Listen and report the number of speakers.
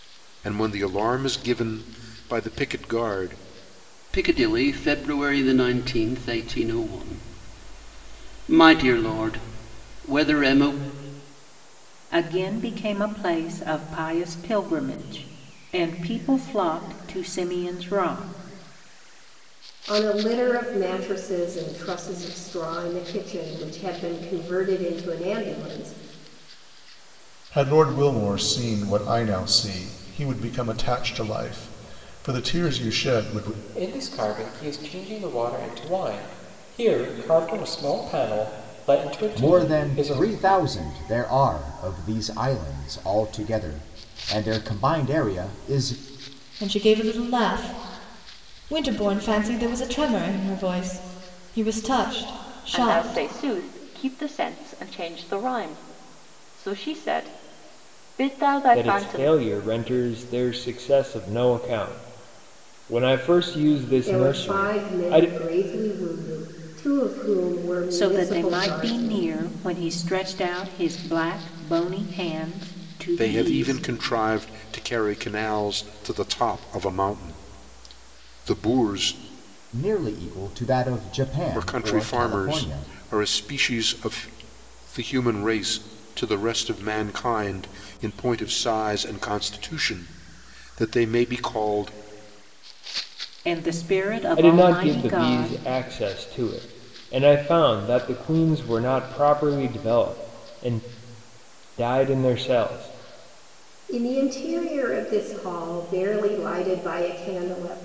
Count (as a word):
ten